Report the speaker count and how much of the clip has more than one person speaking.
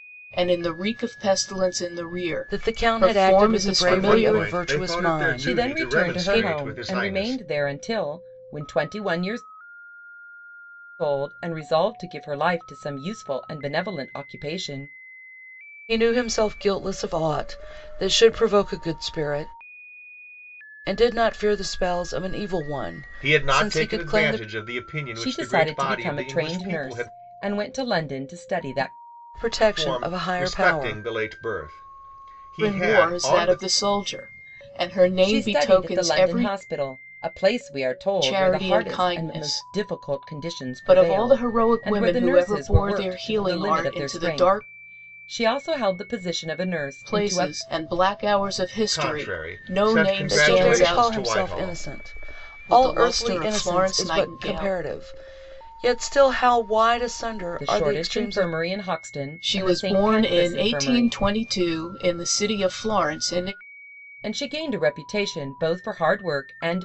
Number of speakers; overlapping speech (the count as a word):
four, about 39%